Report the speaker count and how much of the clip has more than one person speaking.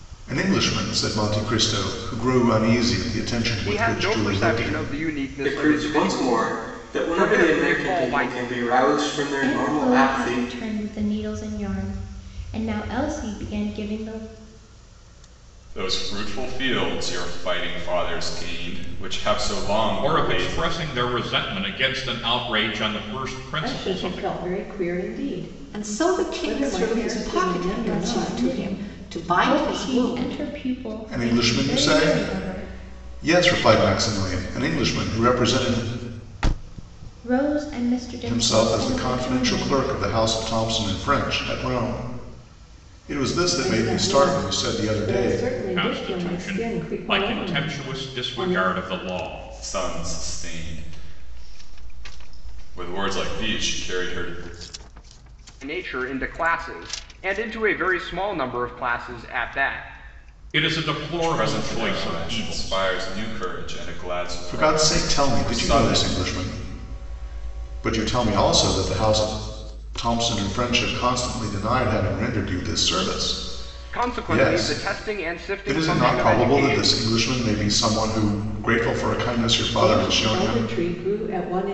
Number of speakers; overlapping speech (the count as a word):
eight, about 32%